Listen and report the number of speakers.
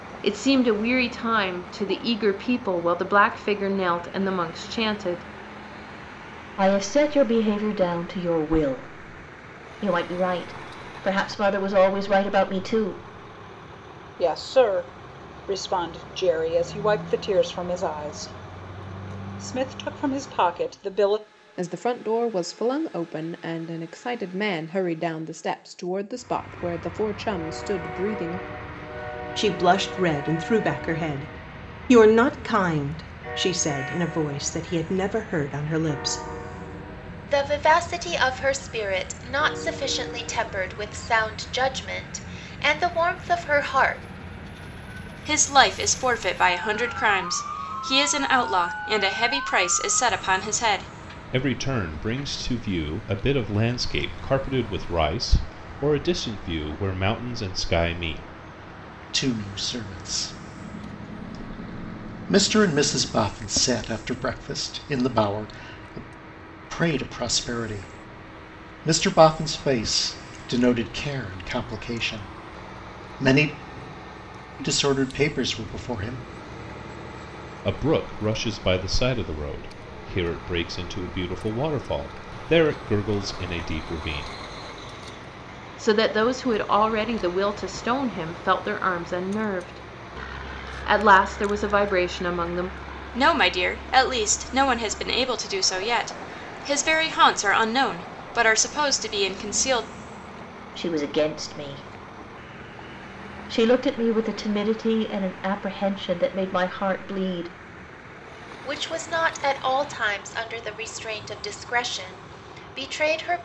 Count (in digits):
9